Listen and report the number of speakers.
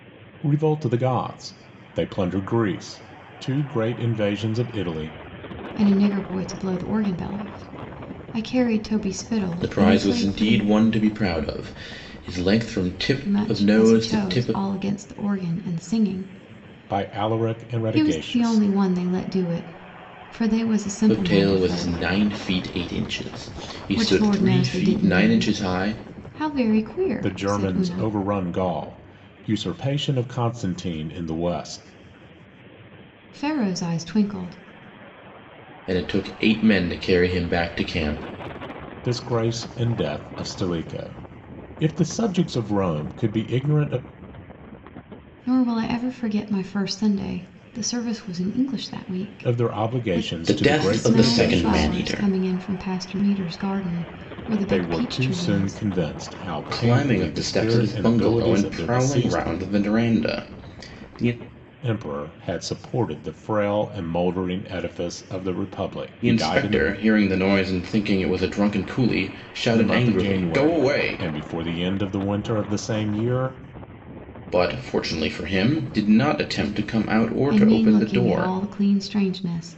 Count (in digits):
3